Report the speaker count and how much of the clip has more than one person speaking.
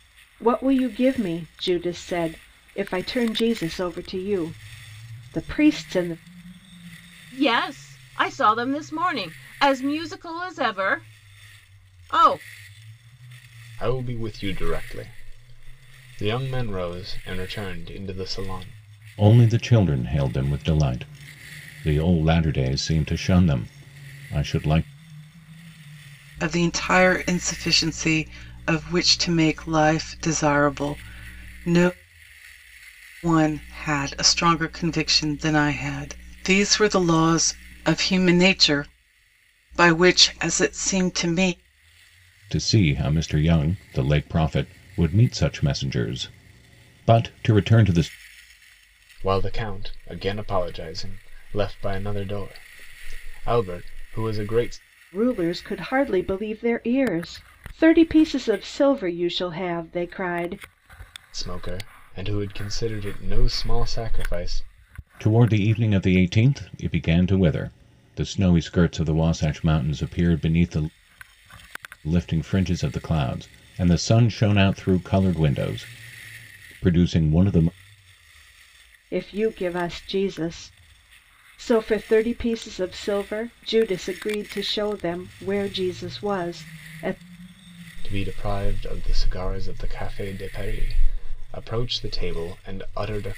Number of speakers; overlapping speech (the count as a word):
five, no overlap